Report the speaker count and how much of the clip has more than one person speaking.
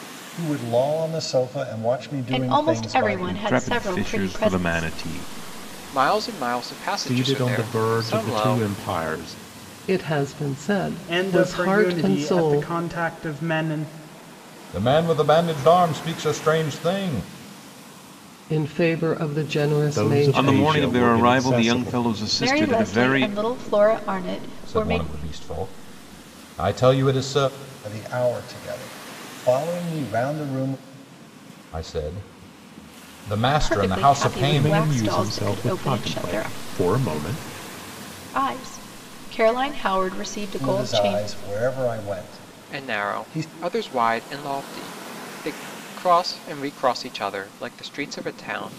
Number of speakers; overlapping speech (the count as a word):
eight, about 29%